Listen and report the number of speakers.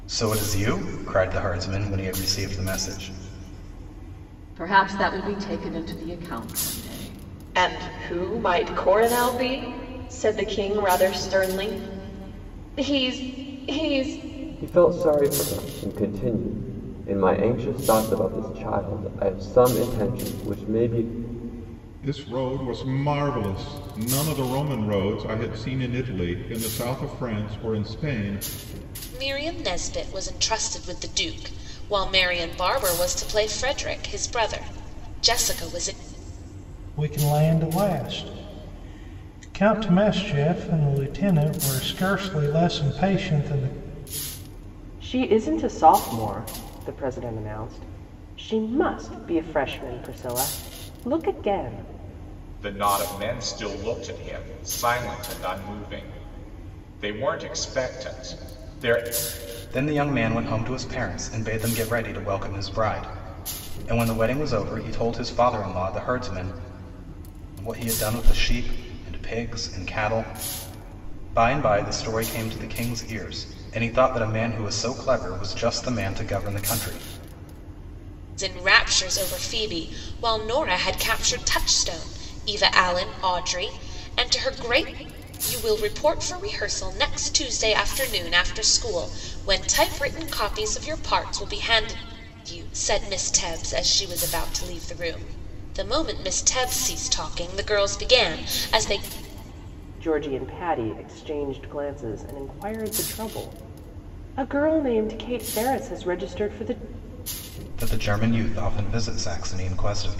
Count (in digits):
9